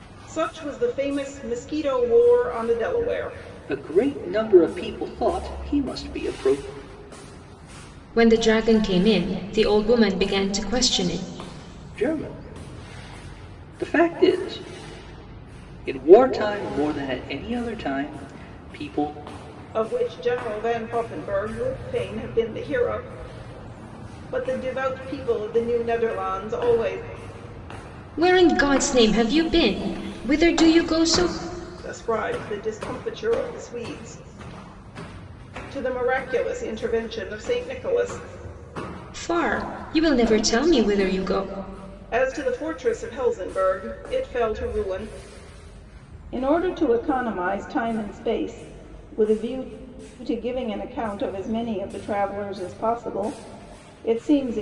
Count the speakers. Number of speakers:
three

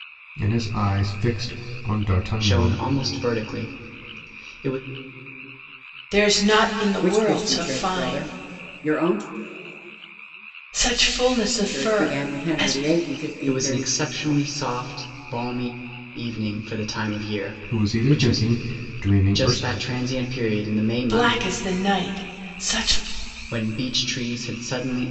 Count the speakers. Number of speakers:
four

